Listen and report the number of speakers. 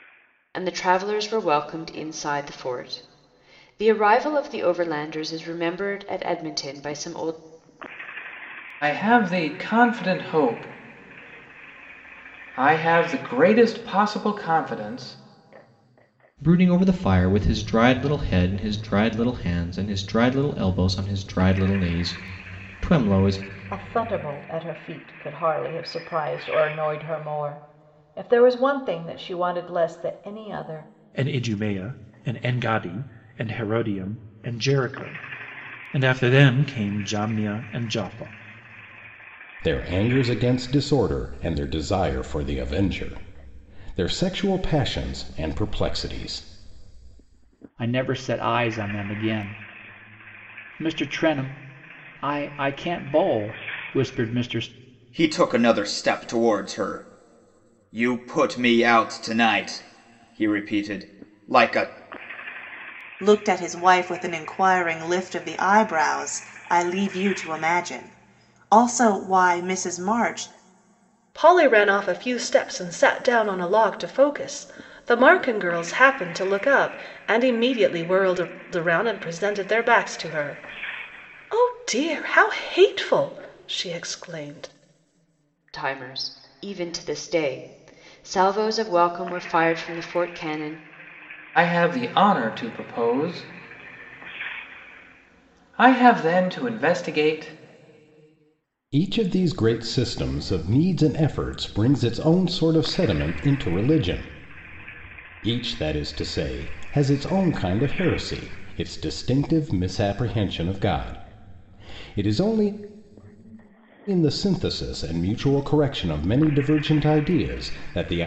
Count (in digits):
10